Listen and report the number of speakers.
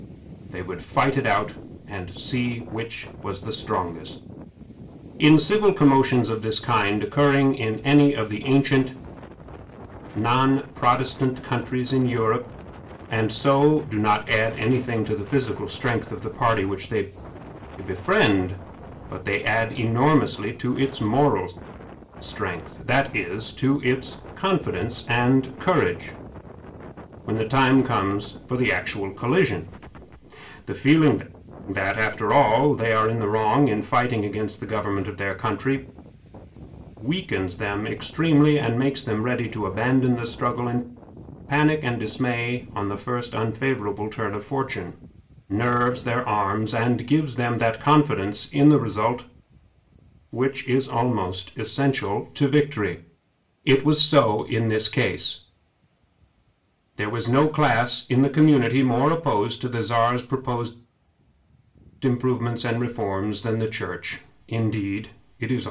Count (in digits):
1